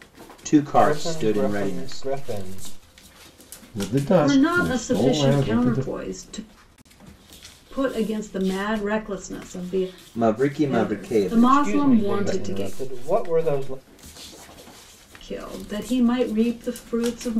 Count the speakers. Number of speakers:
four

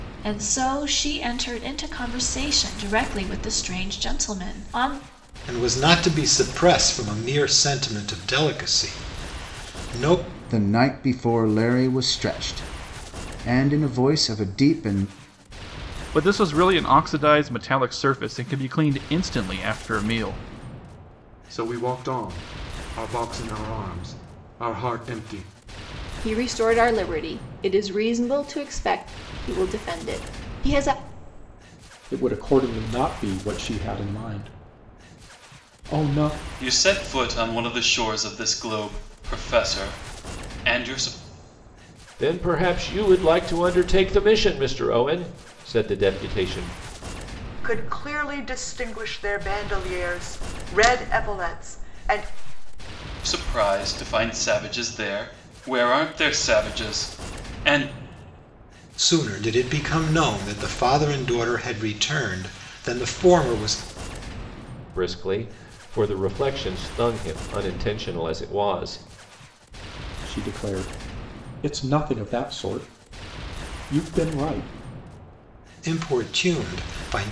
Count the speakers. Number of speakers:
ten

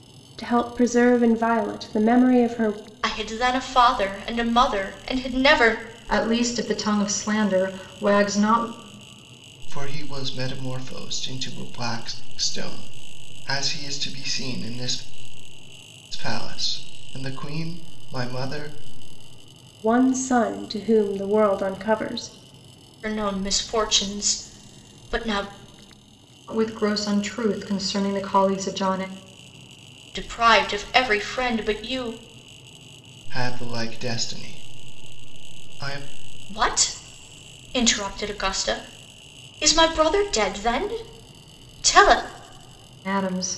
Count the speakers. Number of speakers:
four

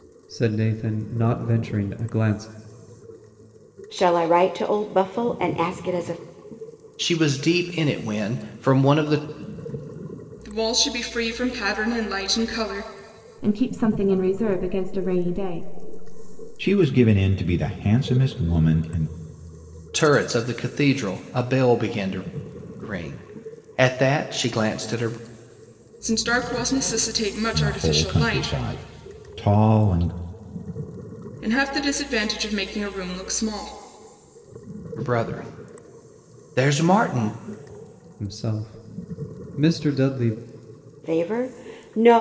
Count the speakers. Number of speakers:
six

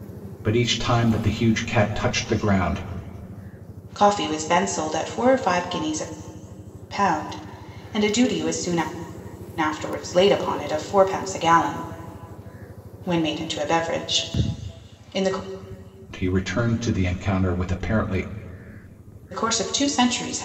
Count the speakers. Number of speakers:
two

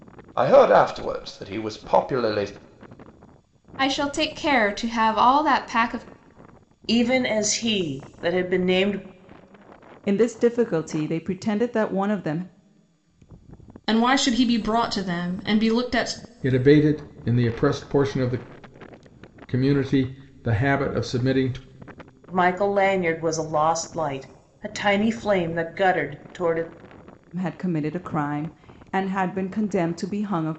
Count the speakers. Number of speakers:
six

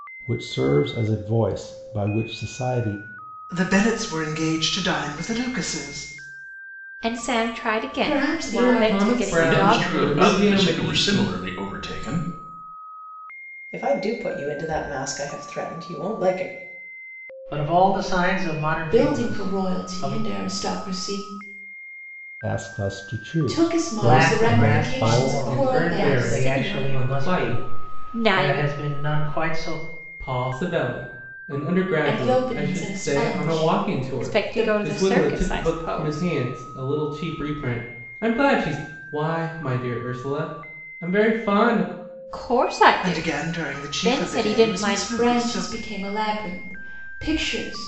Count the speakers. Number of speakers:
eight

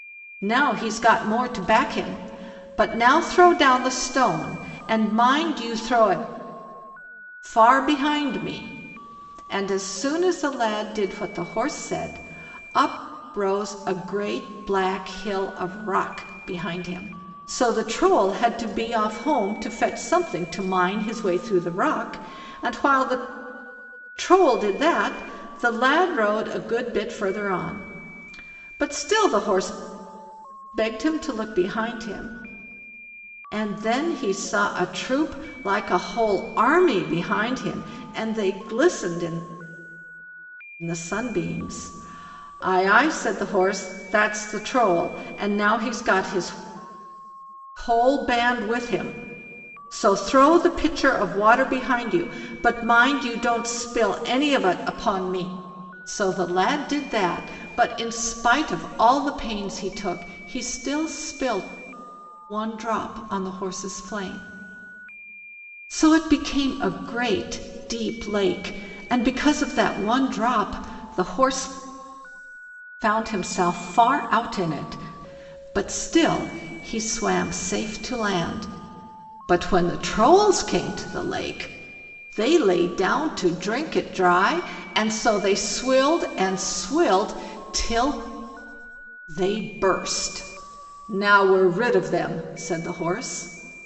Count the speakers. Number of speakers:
one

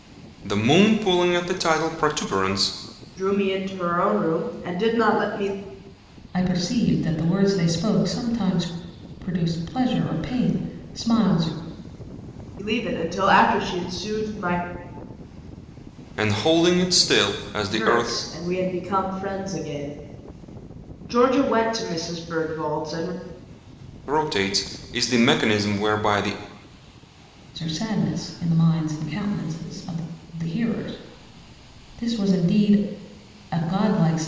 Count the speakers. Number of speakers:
three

